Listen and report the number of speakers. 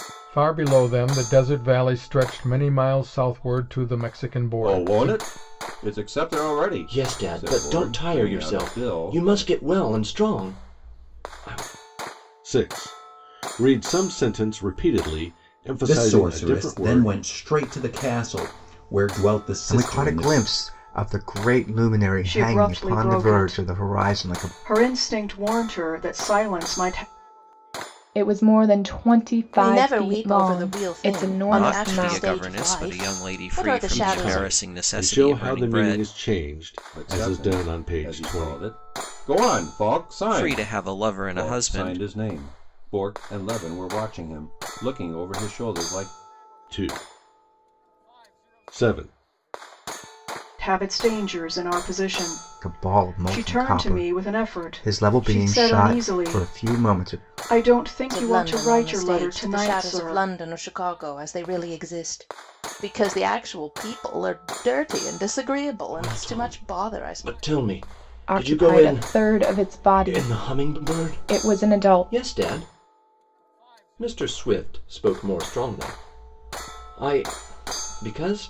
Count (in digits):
10